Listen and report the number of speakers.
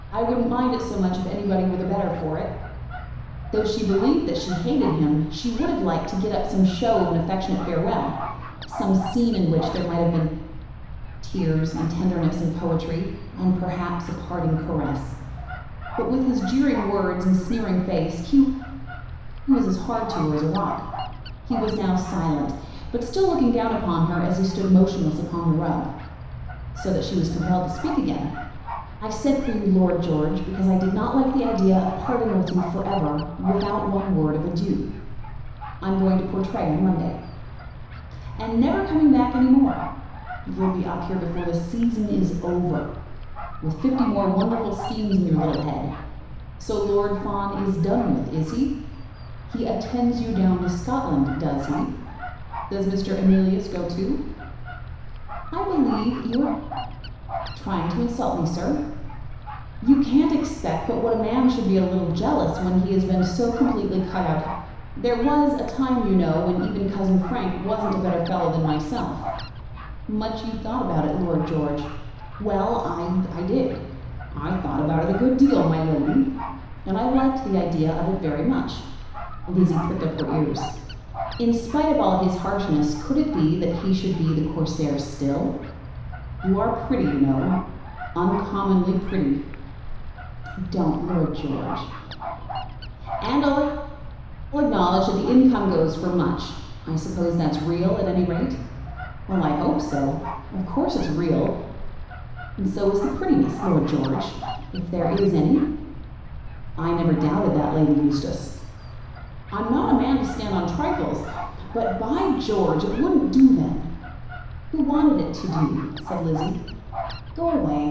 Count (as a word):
one